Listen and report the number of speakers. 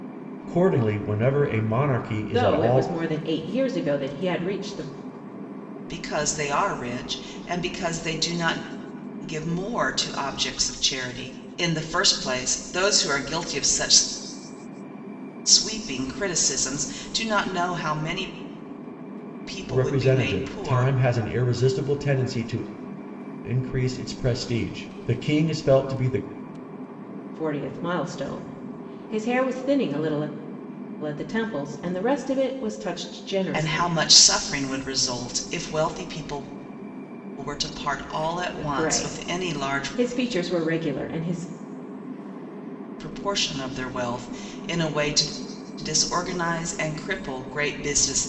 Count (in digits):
3